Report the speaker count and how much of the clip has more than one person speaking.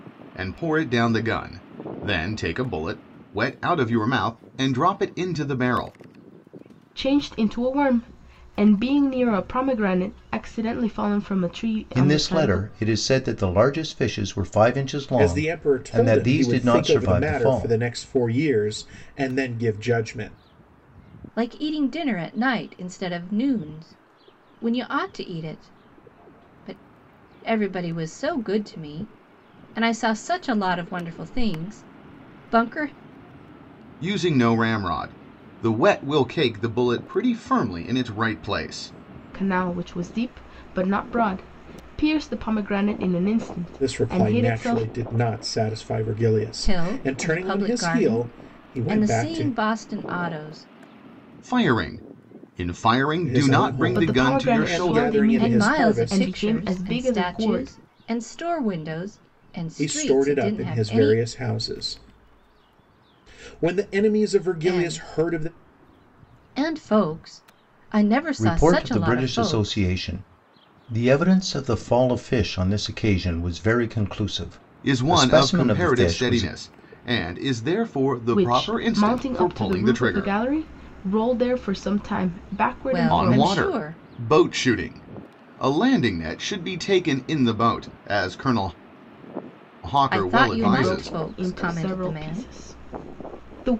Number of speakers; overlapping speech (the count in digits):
5, about 25%